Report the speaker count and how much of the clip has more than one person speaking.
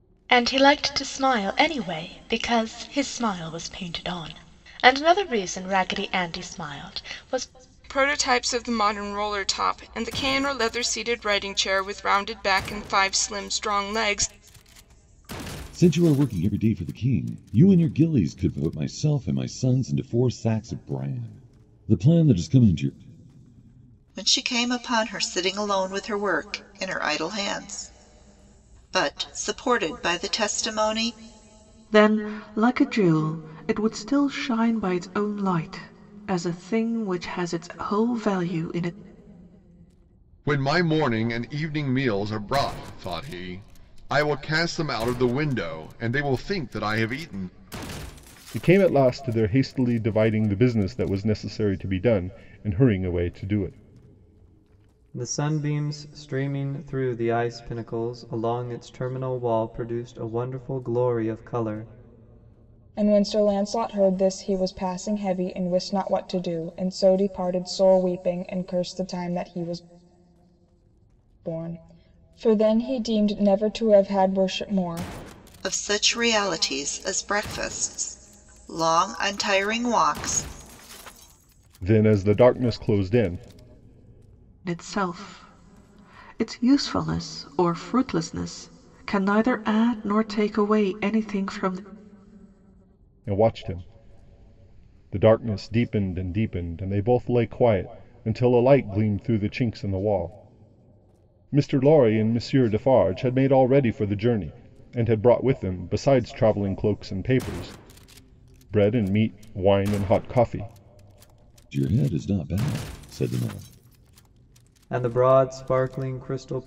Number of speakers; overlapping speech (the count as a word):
nine, no overlap